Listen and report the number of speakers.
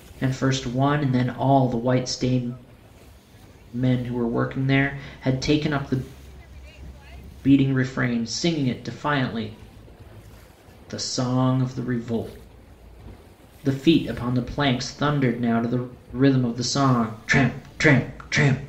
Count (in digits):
1